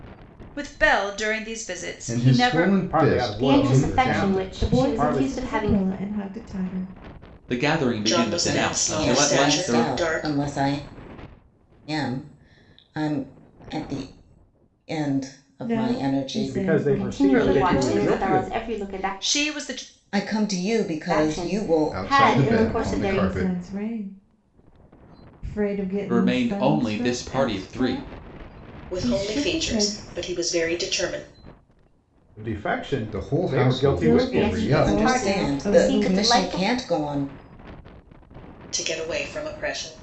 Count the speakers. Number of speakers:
eight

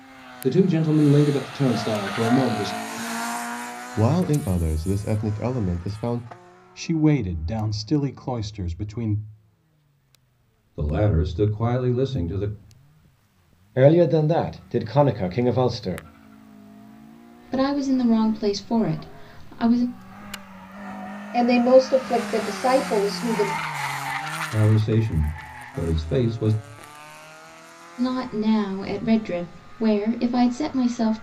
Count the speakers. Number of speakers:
seven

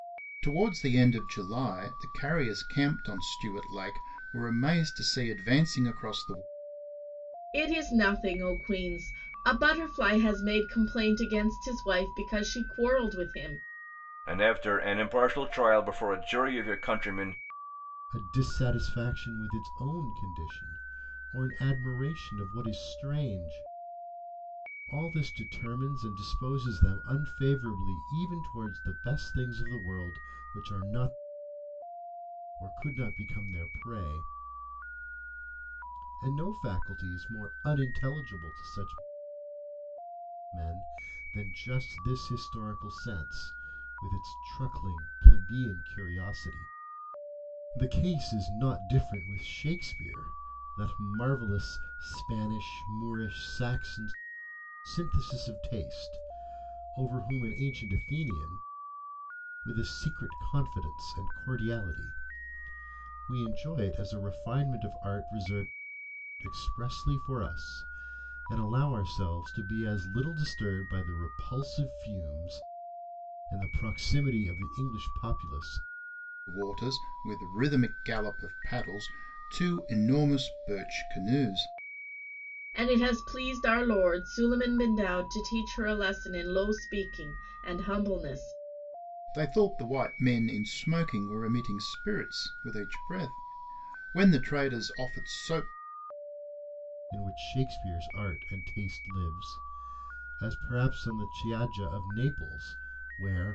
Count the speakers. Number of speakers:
four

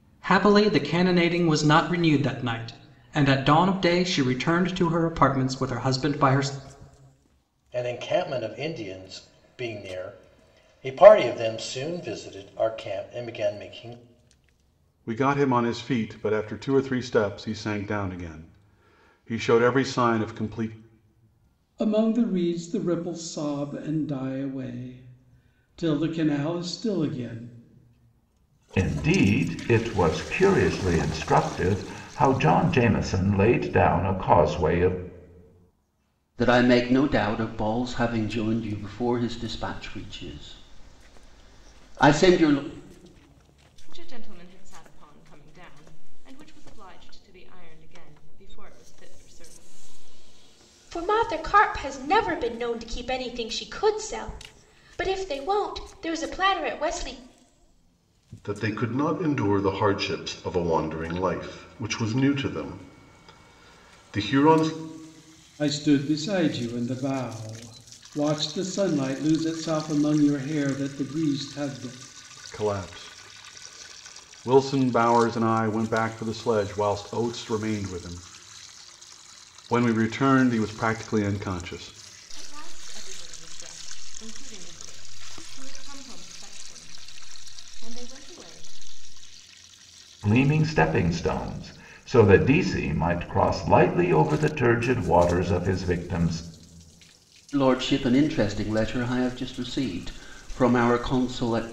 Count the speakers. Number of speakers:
nine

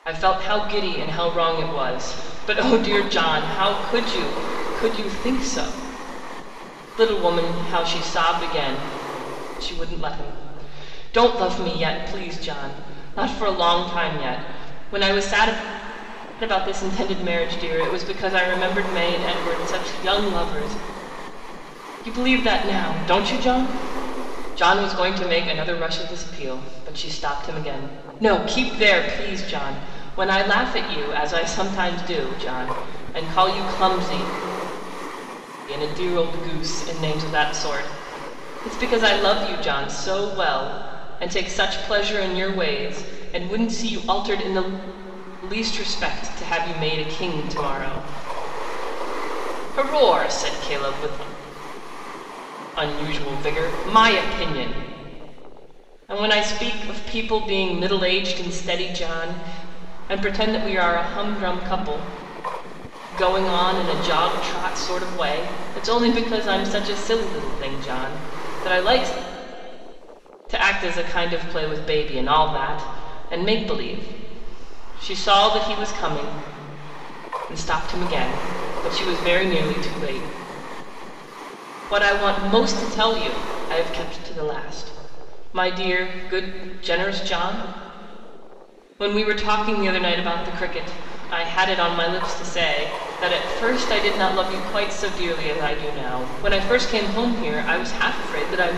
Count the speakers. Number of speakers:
one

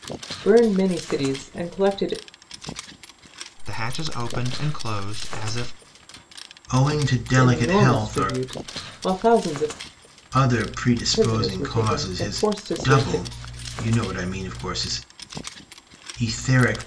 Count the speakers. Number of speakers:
three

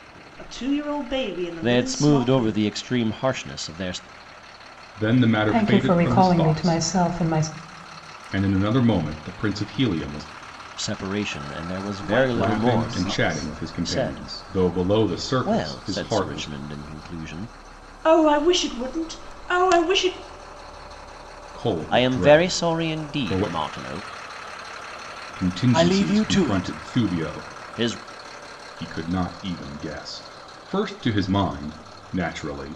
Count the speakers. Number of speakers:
four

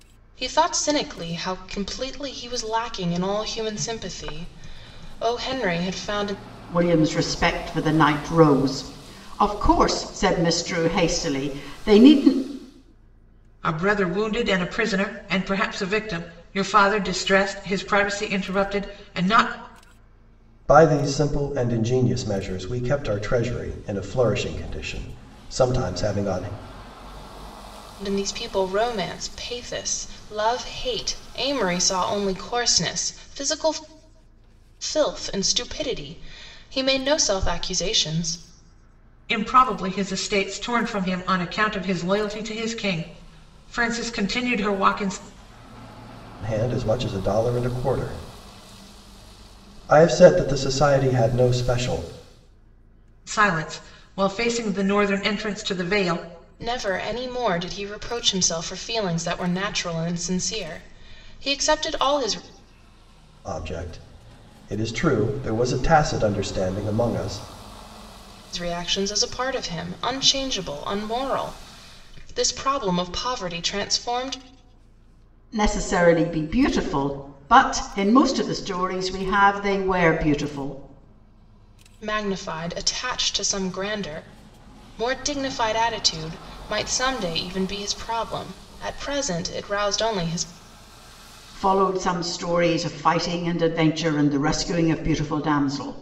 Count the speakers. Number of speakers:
four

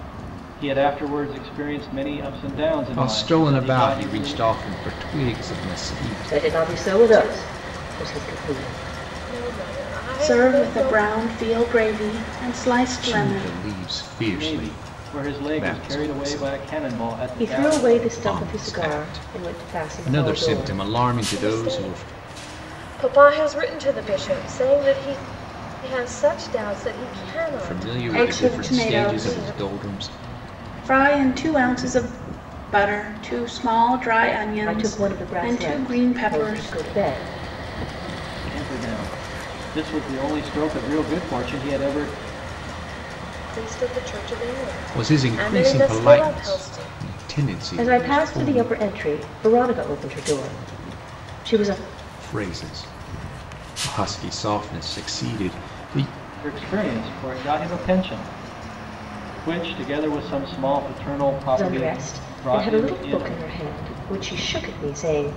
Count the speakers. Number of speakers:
five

